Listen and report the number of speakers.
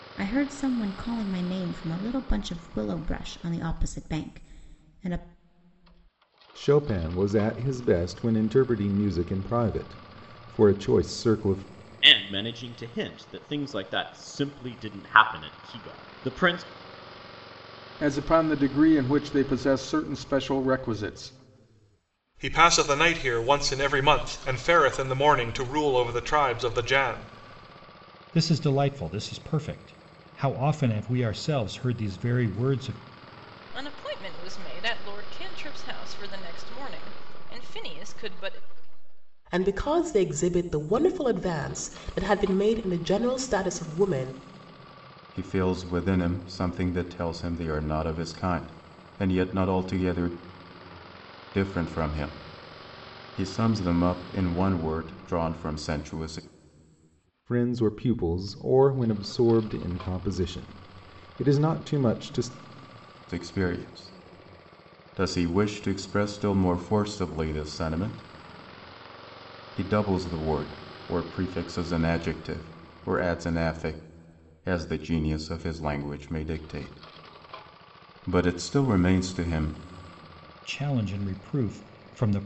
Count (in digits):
9